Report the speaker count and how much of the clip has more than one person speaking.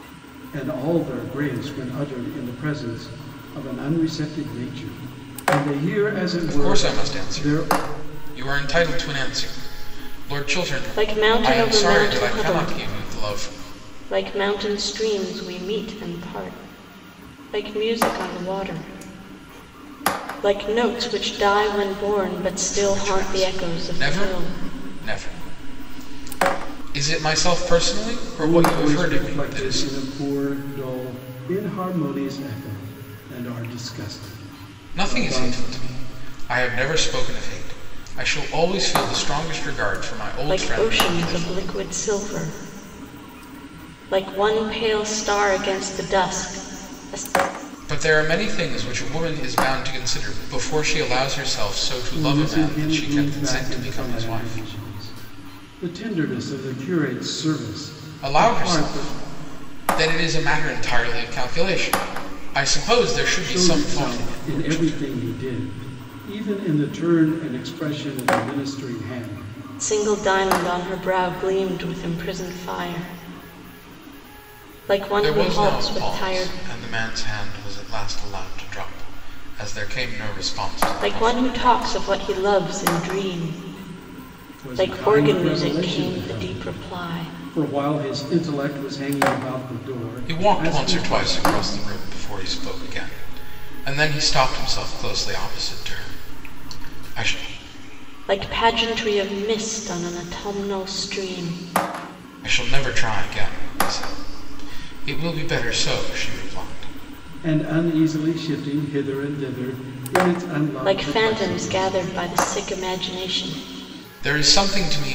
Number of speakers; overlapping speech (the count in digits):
3, about 20%